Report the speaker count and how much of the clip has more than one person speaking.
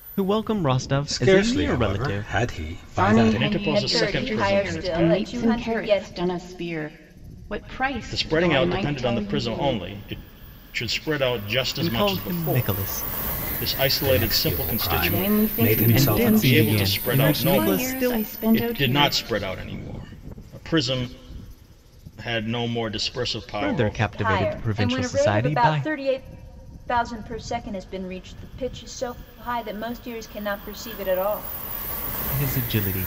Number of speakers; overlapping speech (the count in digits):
5, about 45%